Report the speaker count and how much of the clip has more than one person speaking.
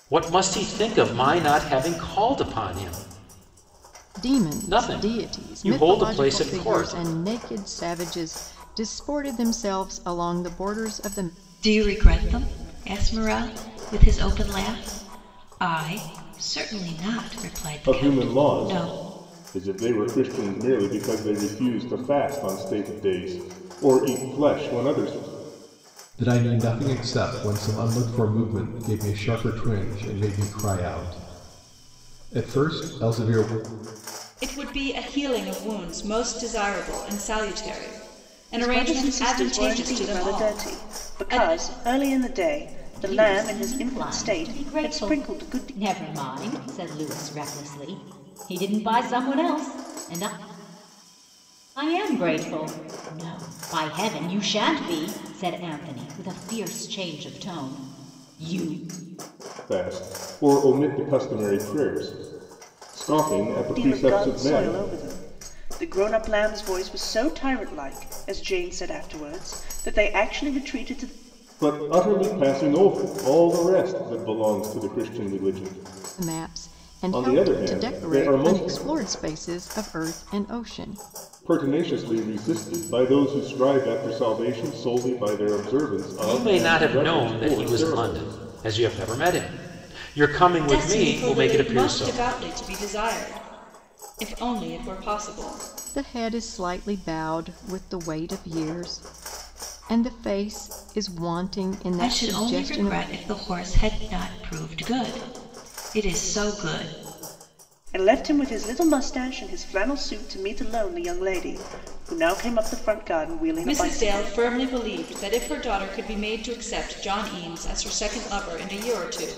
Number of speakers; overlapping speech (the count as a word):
eight, about 16%